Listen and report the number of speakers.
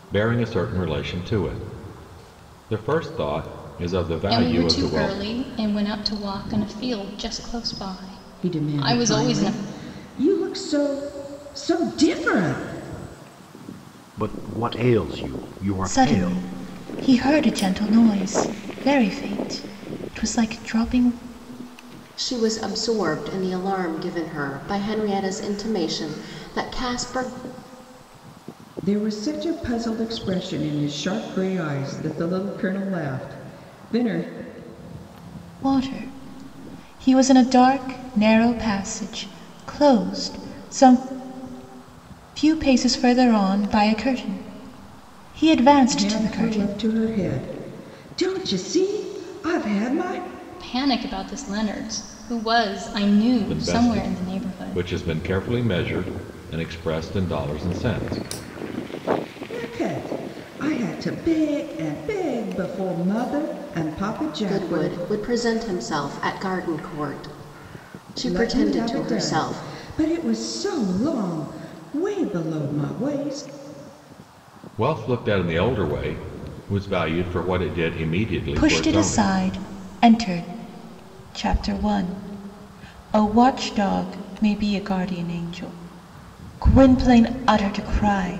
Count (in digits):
6